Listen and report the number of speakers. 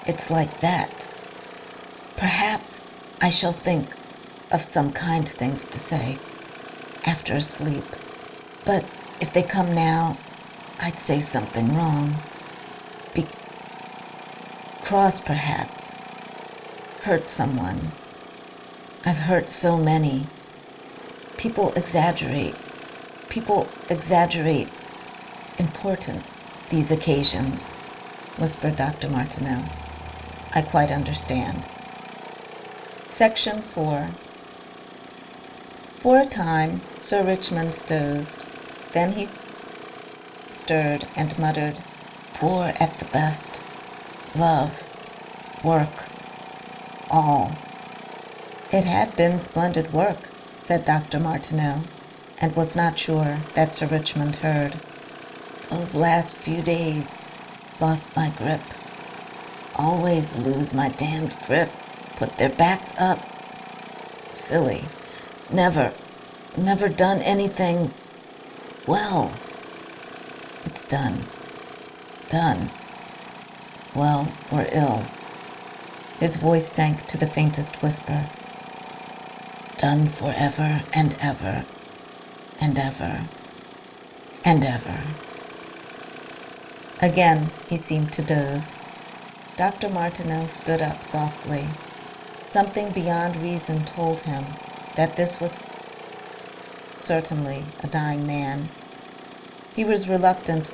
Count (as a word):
one